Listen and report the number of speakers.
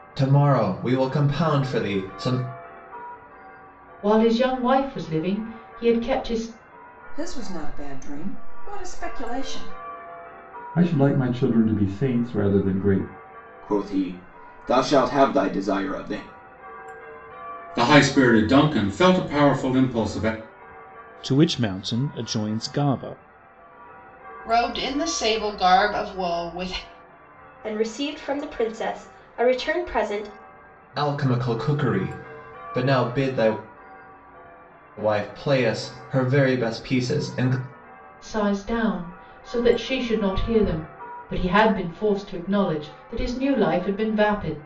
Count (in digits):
9